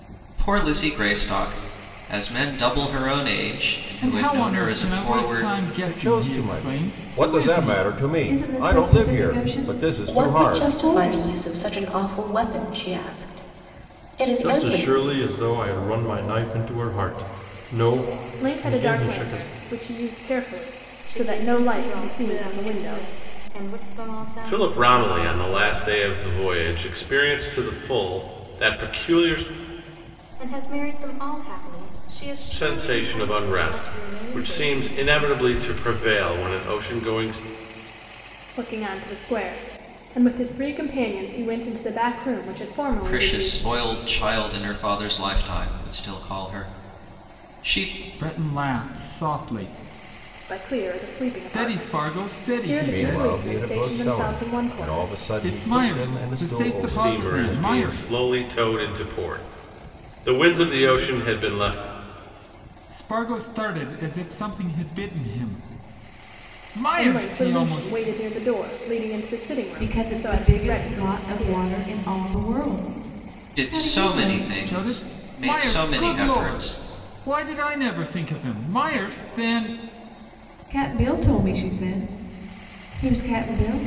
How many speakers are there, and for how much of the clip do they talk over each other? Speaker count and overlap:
nine, about 35%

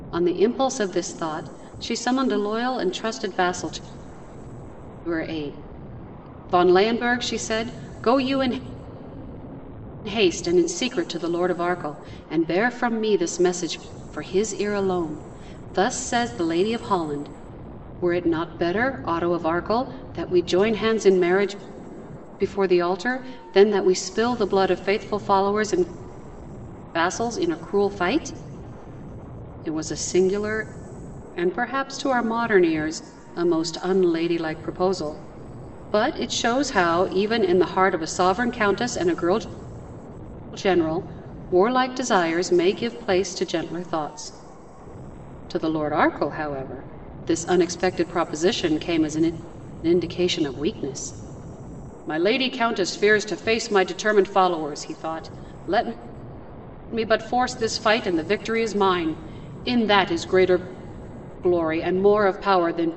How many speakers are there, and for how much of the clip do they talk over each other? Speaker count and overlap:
one, no overlap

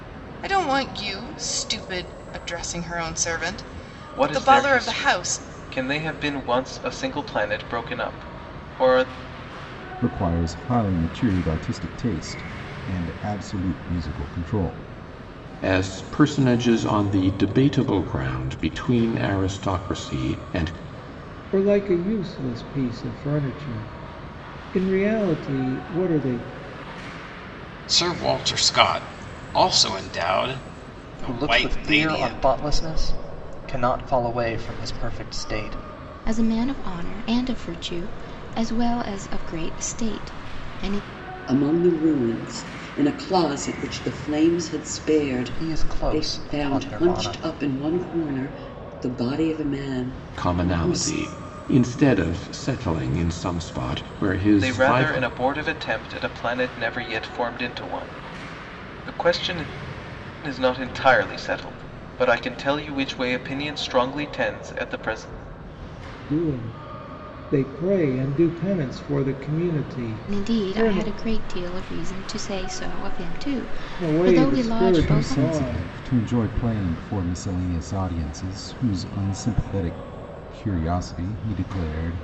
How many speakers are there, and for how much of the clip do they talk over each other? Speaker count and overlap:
nine, about 11%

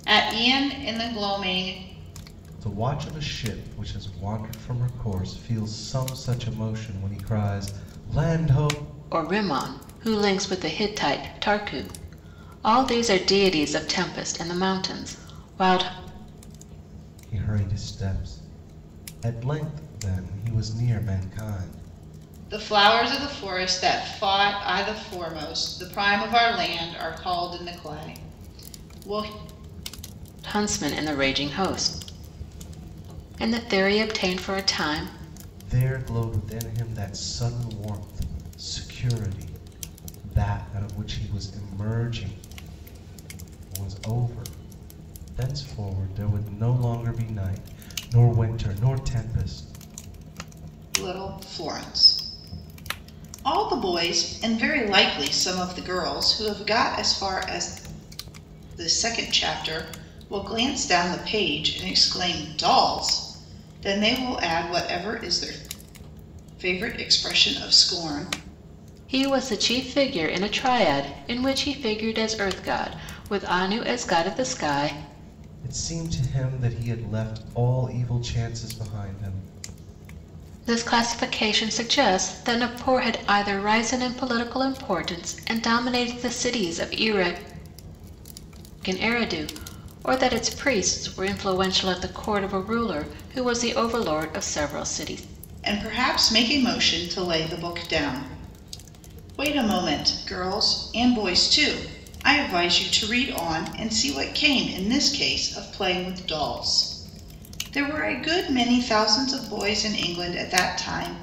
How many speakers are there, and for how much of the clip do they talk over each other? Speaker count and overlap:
three, no overlap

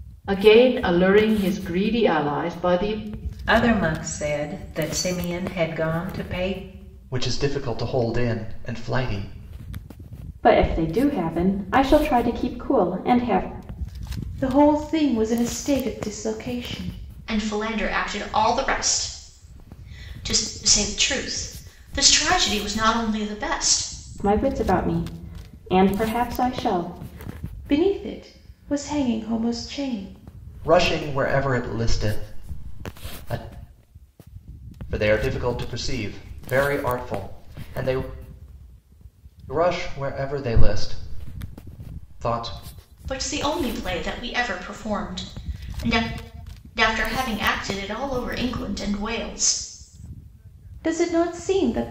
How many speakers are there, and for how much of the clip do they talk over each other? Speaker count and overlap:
six, no overlap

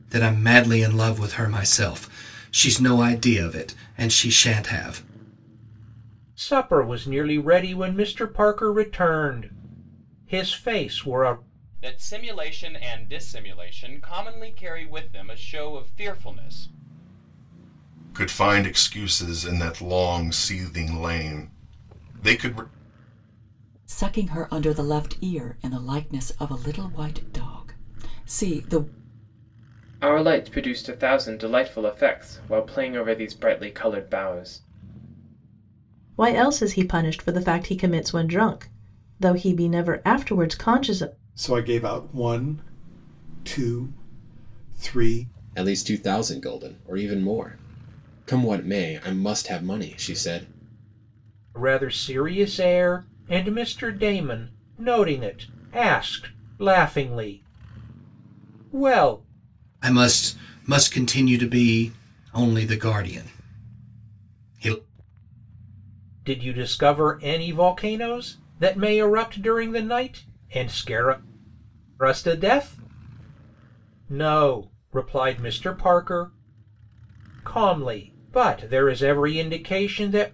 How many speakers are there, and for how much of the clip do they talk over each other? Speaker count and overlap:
nine, no overlap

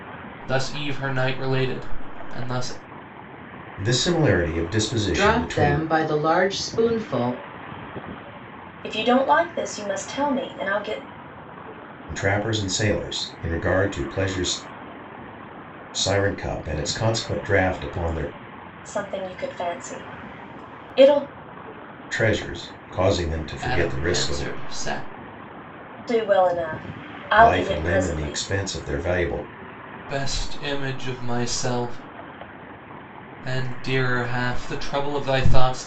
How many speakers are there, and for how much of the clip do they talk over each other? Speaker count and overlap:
four, about 7%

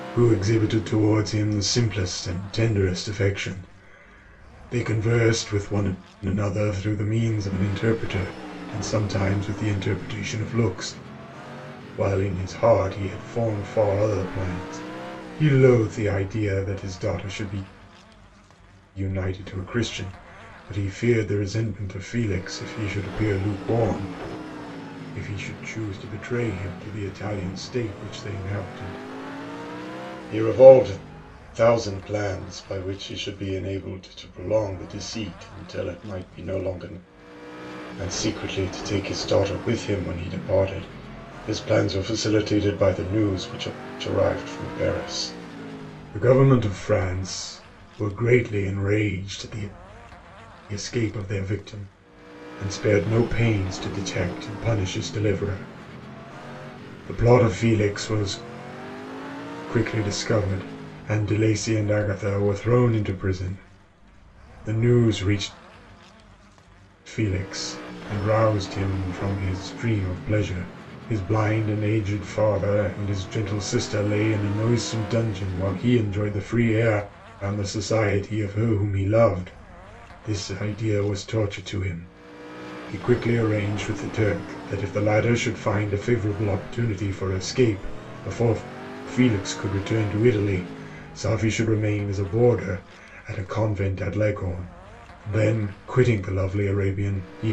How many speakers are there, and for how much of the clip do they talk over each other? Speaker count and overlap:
one, no overlap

